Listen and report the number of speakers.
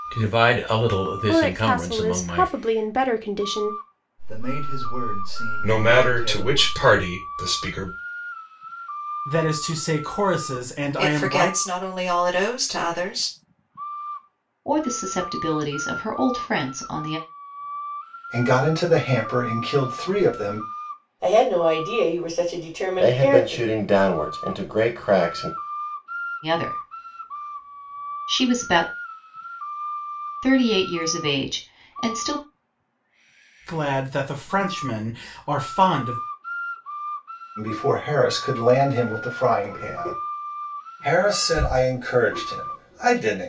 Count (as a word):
ten